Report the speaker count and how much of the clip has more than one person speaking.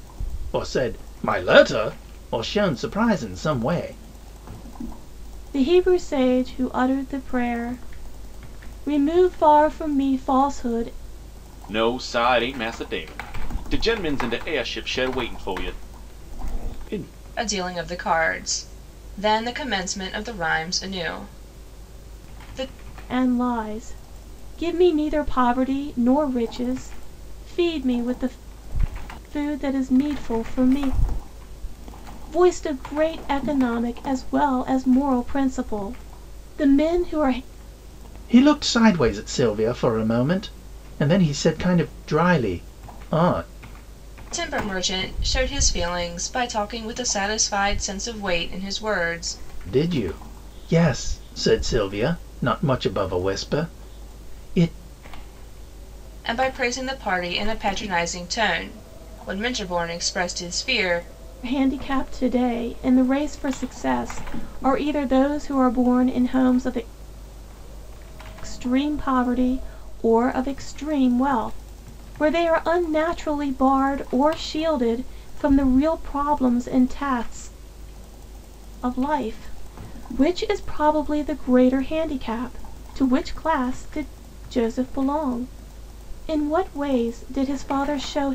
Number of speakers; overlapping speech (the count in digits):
4, no overlap